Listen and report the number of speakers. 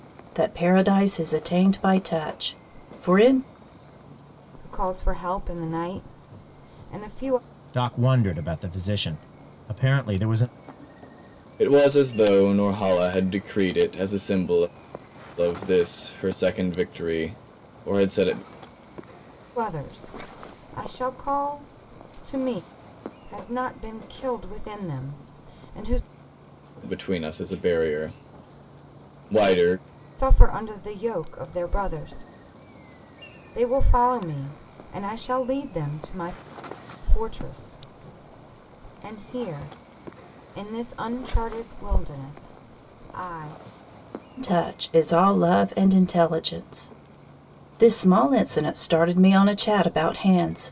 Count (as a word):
four